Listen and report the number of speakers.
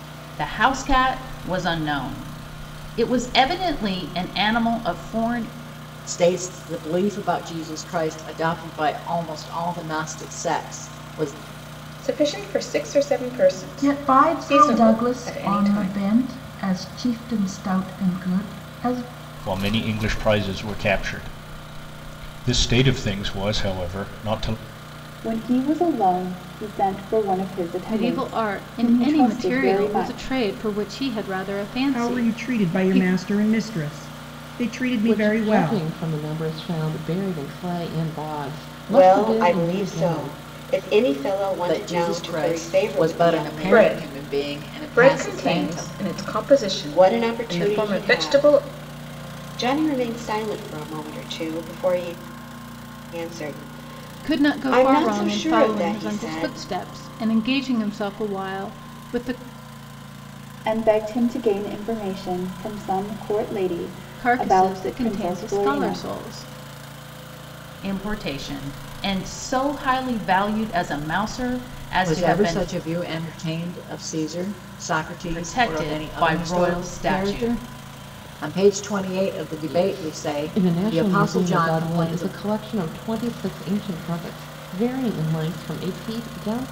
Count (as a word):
ten